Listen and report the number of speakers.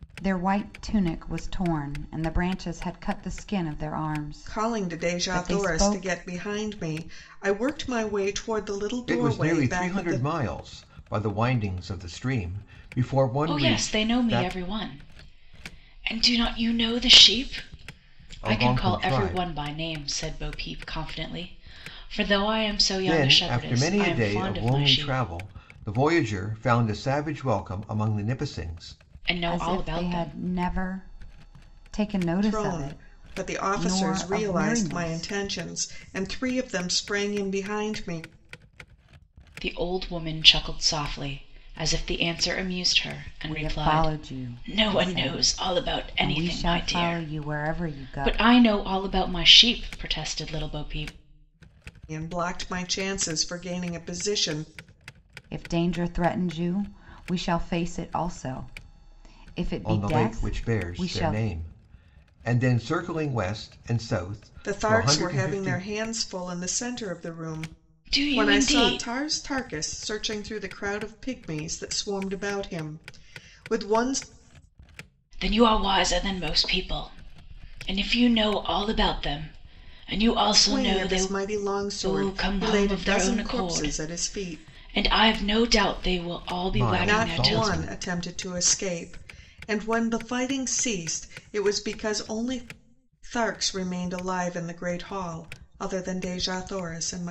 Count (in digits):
4